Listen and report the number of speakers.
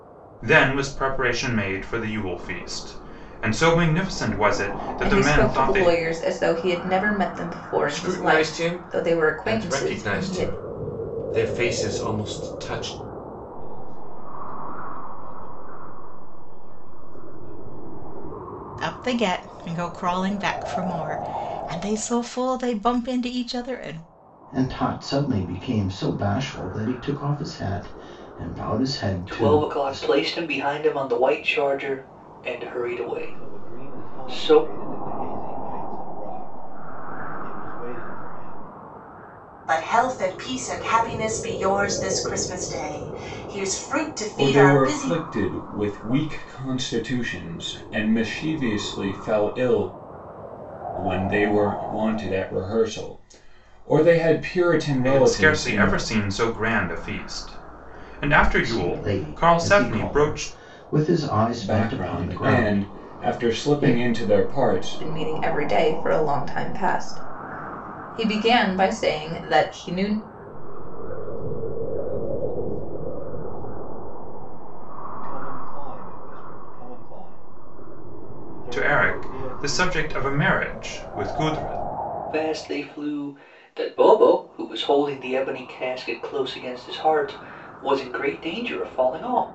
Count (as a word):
ten